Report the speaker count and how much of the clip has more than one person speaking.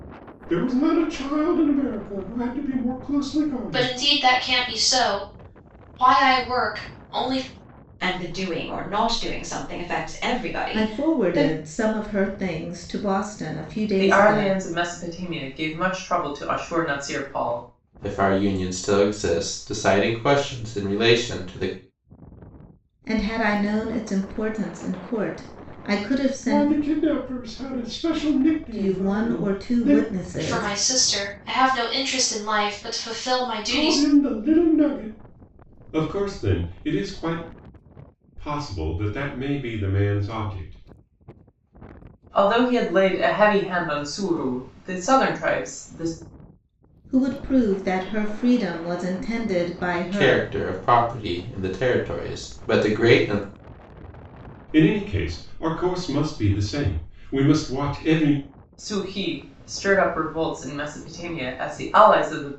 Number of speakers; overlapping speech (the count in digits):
6, about 7%